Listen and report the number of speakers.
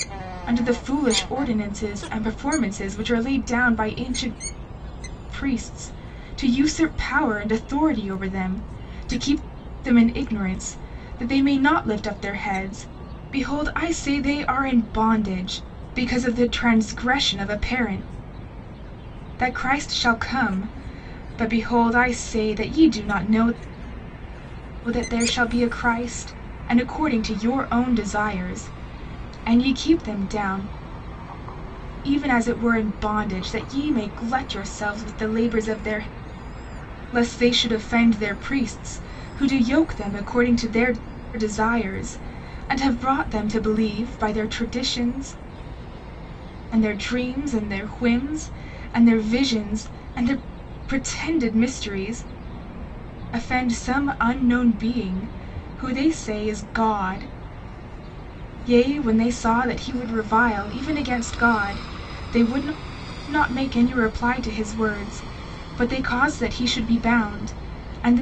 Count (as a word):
one